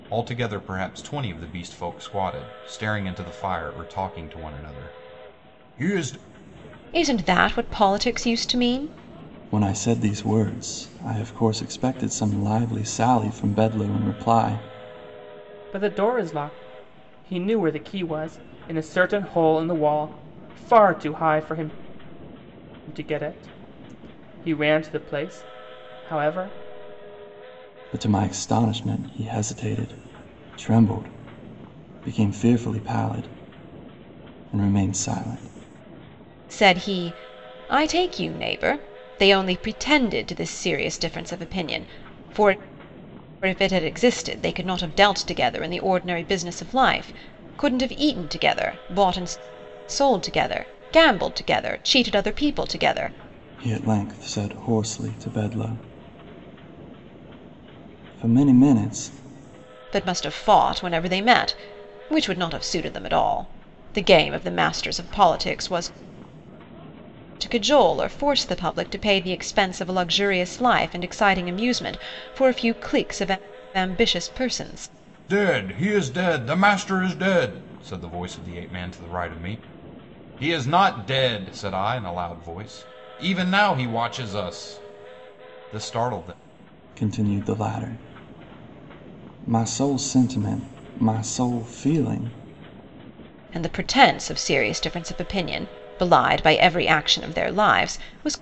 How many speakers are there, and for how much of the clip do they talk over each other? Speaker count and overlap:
4, no overlap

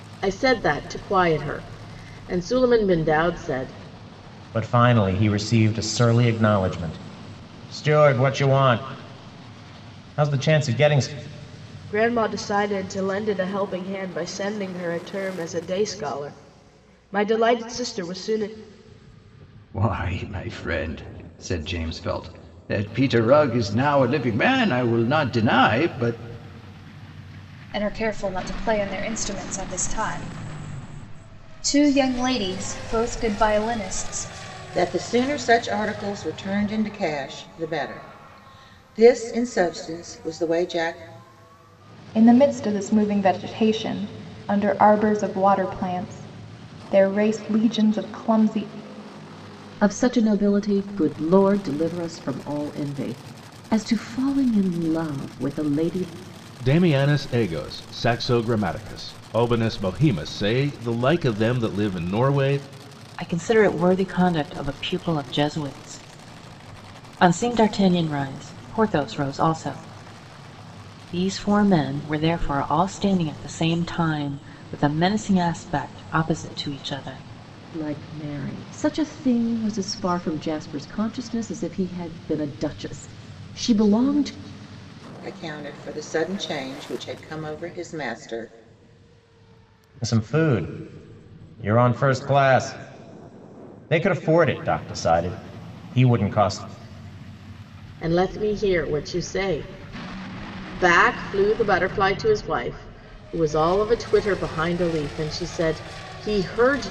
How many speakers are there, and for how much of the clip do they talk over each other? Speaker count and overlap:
10, no overlap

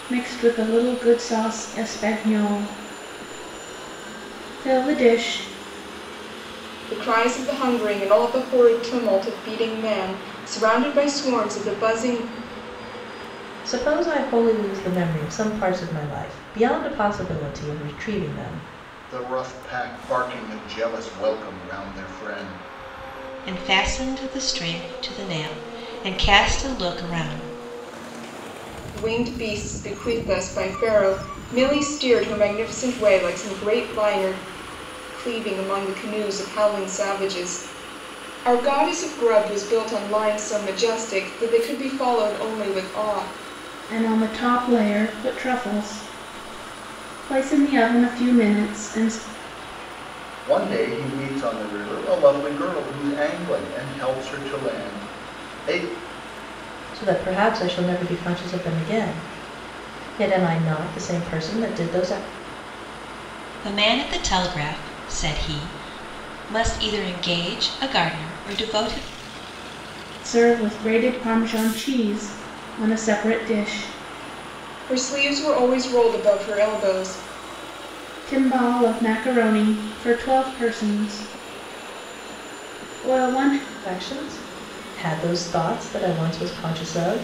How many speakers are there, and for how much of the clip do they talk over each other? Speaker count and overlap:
5, no overlap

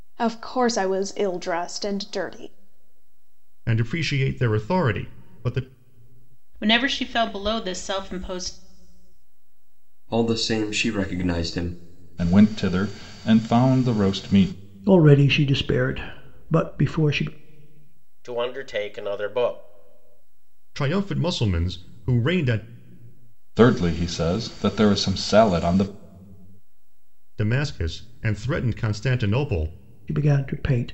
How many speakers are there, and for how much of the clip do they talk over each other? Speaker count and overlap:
7, no overlap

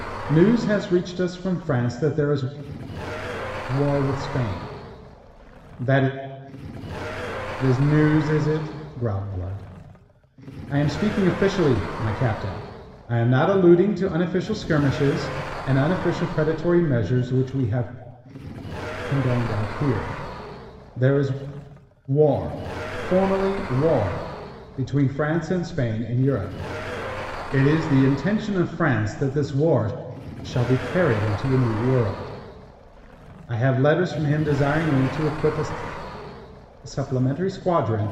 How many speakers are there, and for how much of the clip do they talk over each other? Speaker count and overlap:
1, no overlap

